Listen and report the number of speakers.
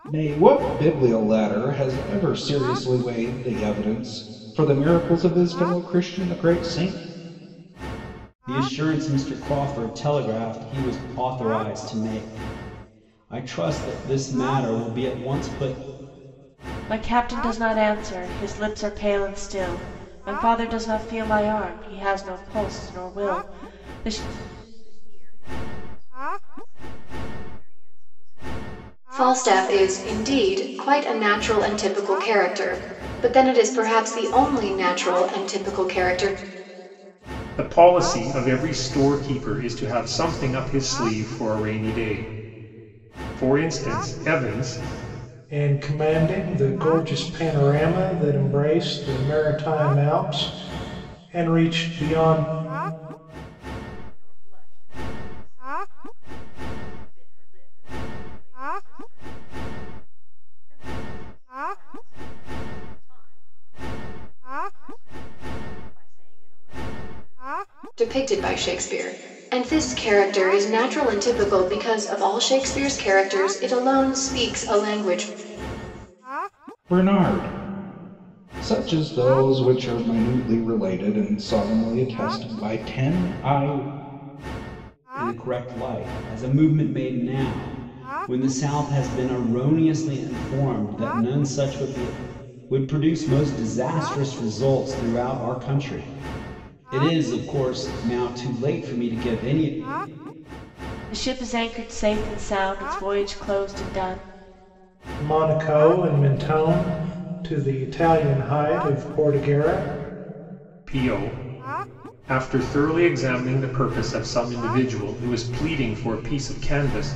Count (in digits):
7